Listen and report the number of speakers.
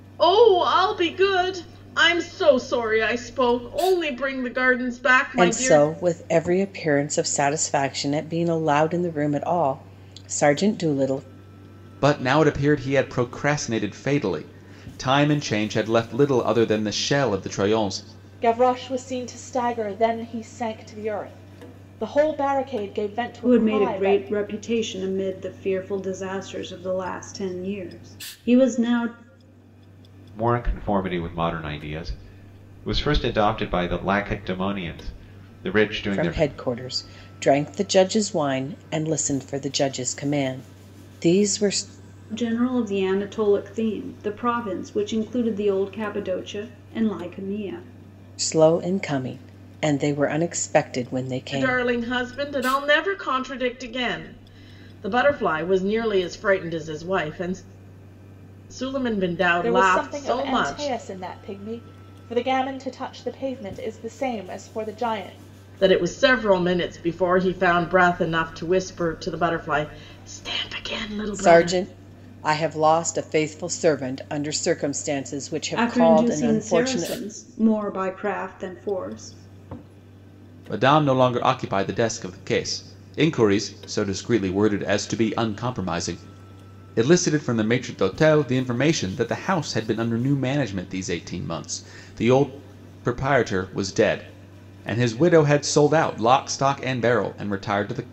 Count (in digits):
6